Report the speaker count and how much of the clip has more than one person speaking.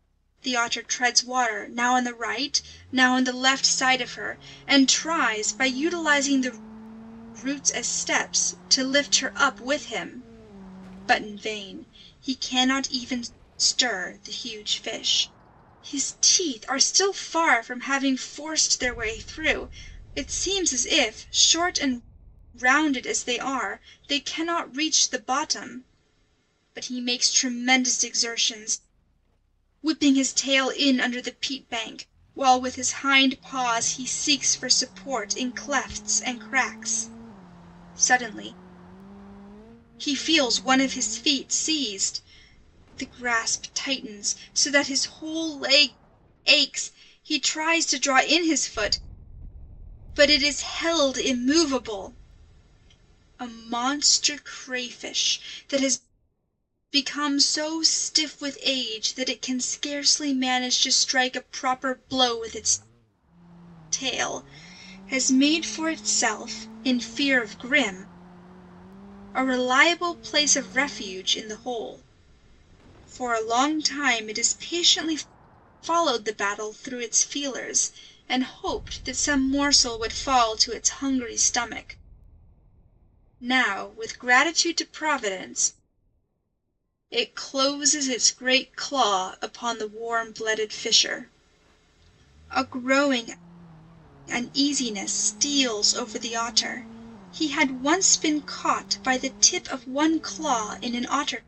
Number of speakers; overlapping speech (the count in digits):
1, no overlap